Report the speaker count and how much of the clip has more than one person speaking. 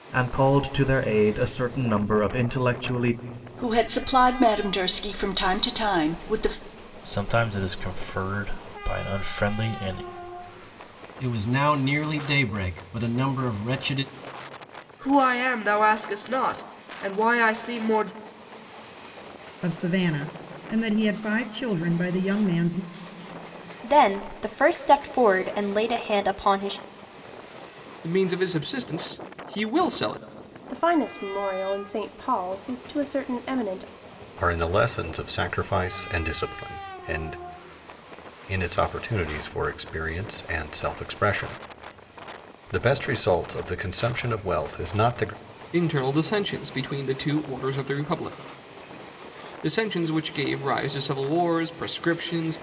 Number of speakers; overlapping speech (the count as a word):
ten, no overlap